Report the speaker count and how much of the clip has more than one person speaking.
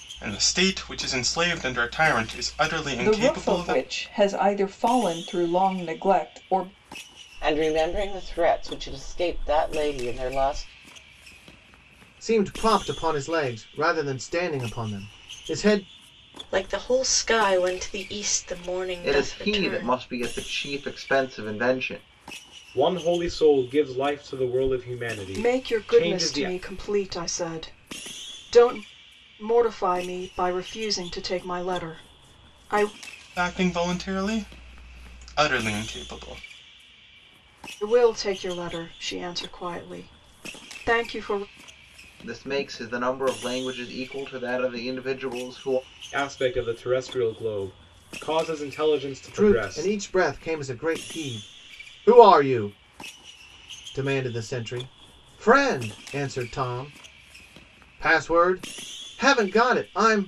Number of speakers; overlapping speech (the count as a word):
eight, about 6%